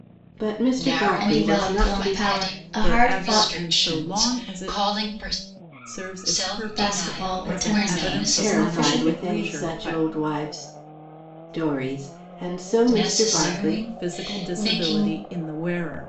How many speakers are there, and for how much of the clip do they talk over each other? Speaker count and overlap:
four, about 62%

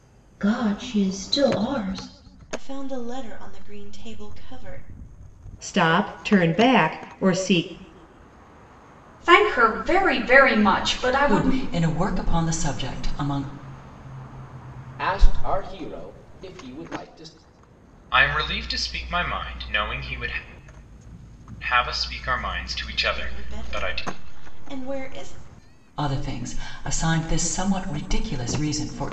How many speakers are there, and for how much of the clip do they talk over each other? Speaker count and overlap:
seven, about 4%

